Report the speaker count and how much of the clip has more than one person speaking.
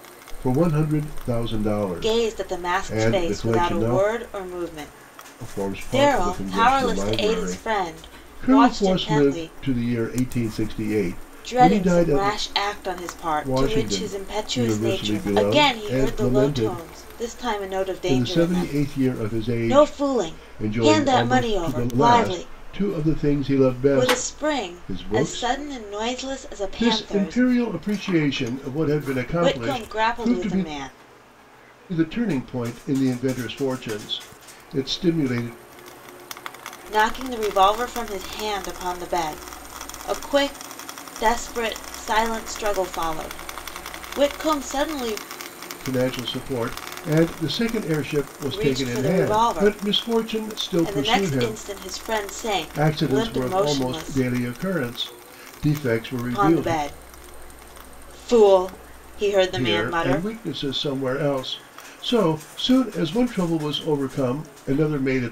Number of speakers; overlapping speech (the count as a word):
two, about 33%